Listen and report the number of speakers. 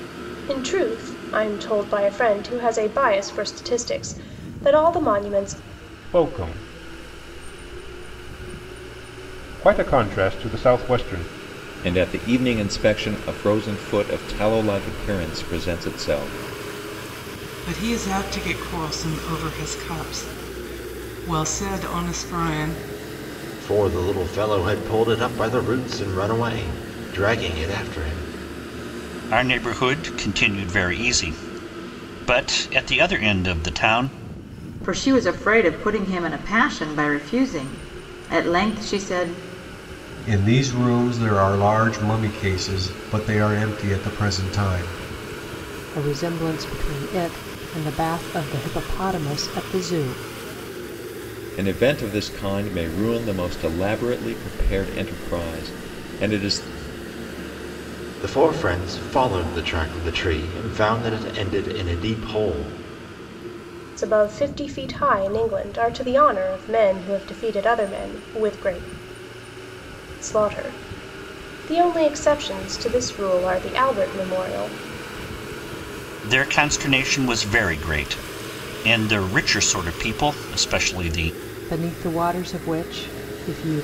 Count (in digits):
9